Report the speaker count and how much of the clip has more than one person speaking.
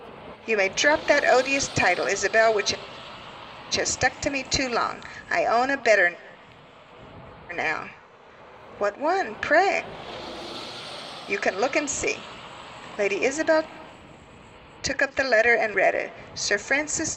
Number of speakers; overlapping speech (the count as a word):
one, no overlap